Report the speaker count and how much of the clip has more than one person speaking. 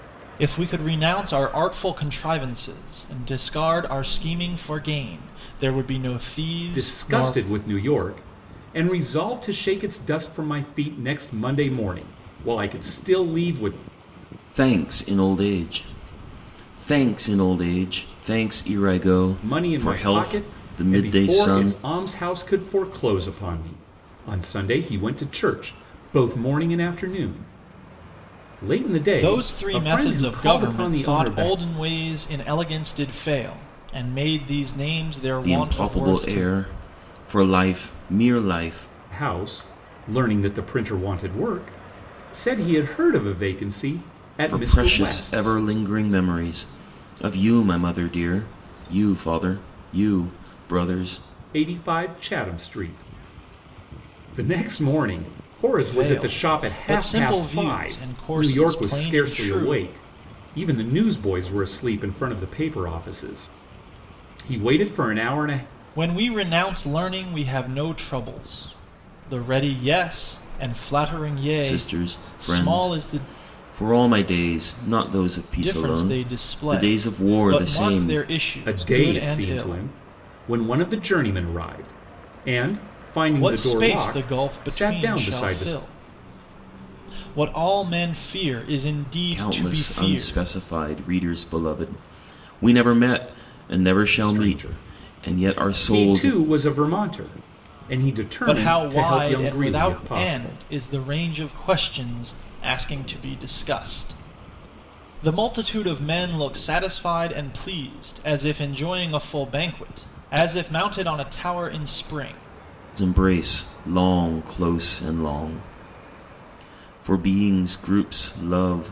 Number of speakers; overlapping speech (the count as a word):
three, about 21%